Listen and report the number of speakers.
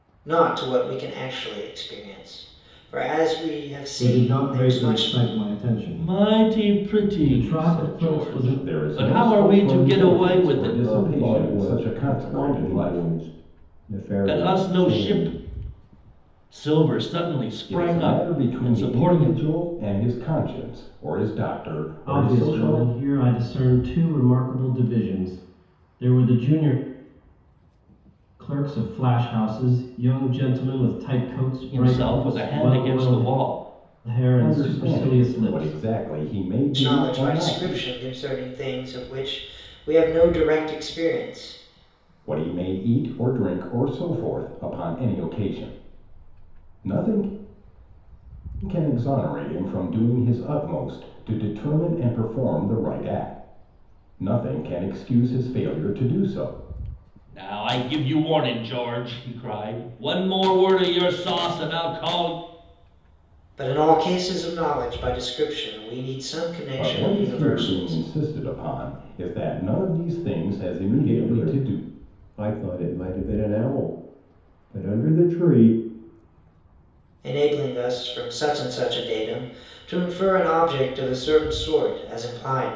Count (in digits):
5